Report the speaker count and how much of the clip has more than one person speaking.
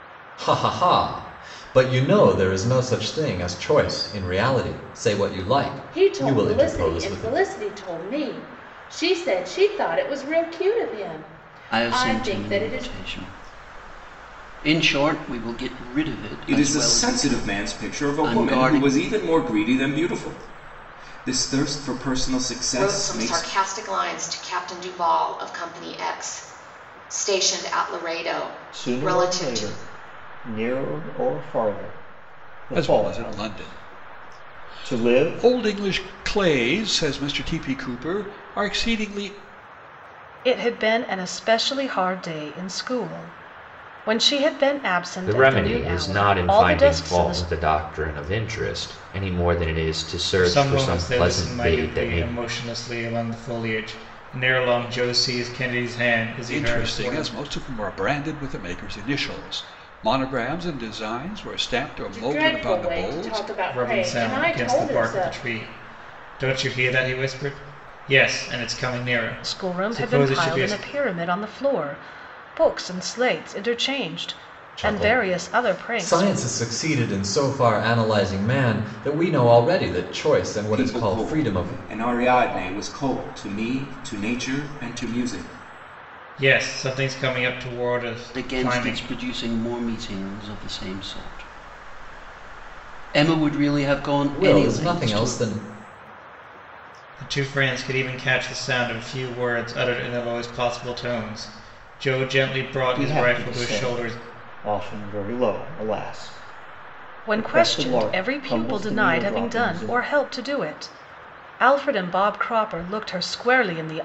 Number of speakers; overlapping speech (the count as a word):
ten, about 24%